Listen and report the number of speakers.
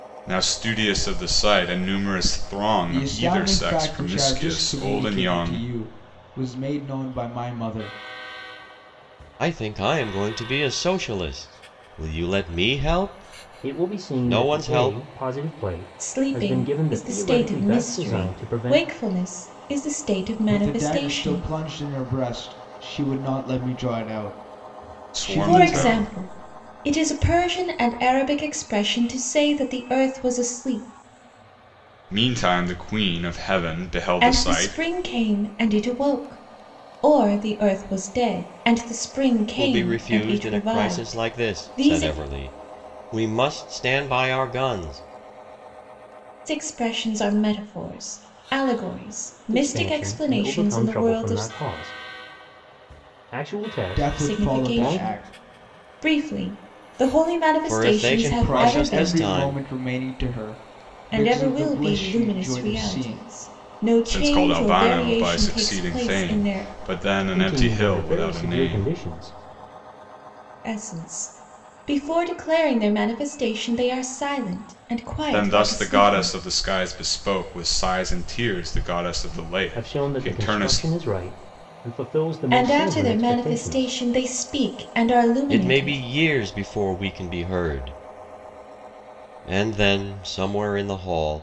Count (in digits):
5